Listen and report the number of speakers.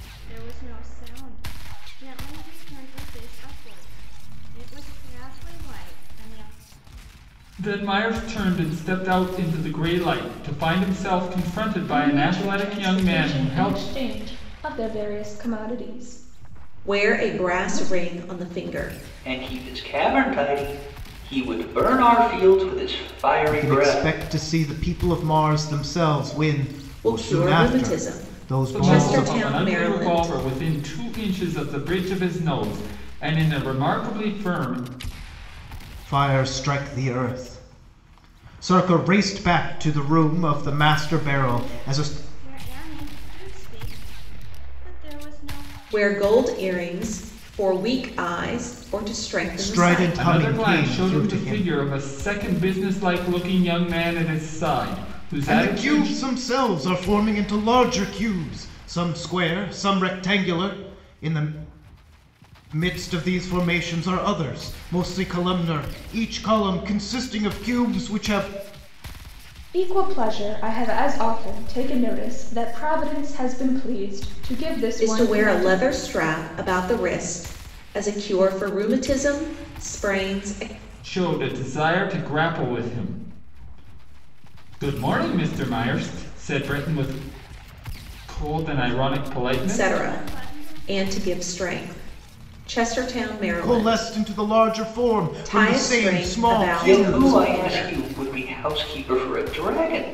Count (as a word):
six